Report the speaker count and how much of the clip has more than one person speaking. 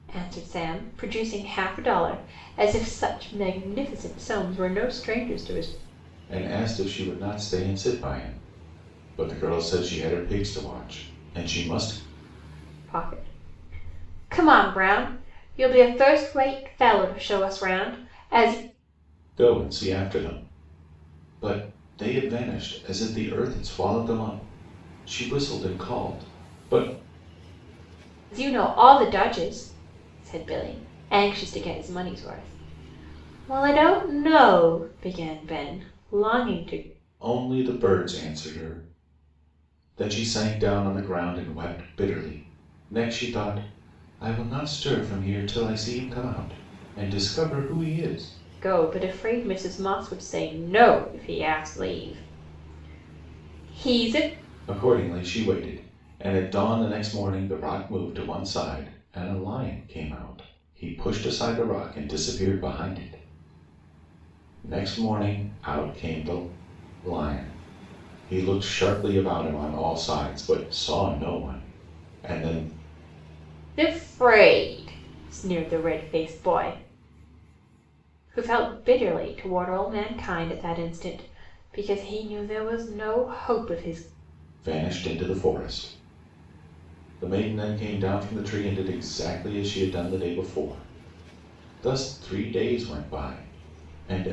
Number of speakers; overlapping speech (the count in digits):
2, no overlap